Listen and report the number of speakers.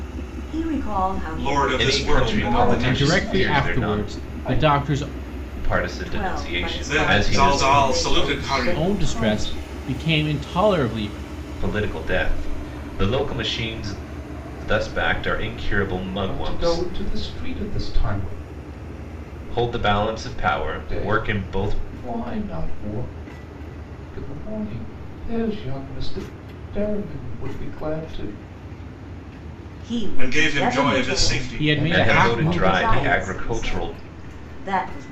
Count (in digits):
5